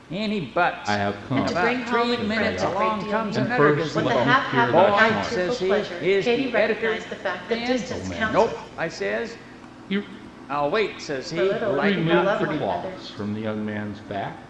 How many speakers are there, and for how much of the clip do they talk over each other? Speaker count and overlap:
3, about 68%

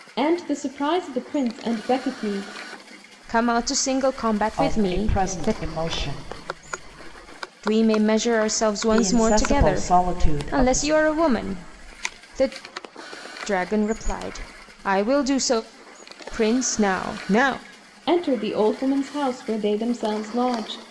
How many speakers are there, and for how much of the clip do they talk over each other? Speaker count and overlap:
3, about 12%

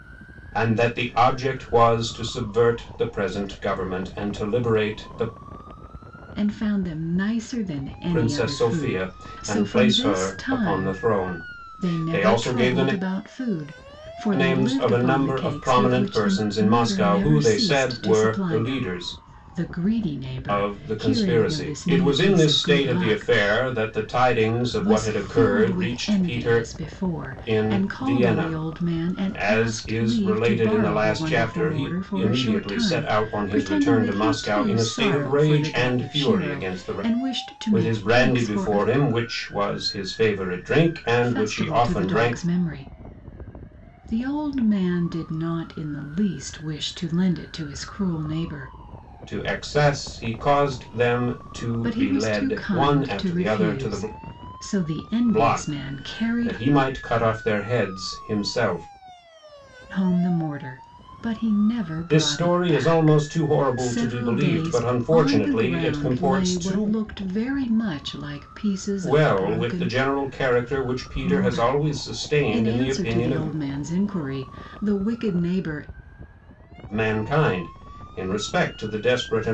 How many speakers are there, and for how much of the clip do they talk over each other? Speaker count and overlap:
2, about 46%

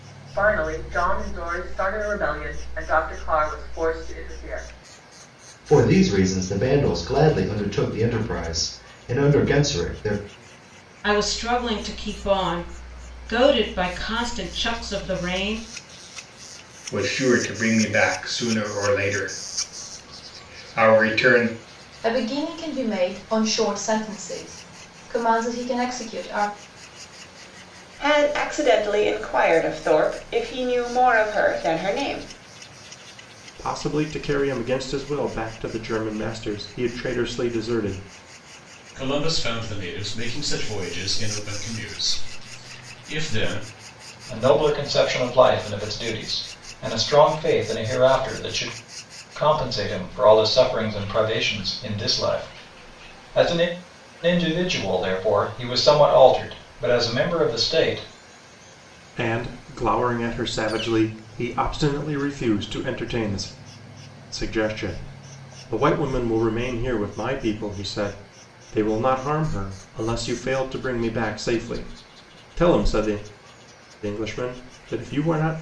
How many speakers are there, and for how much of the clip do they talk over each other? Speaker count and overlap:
9, no overlap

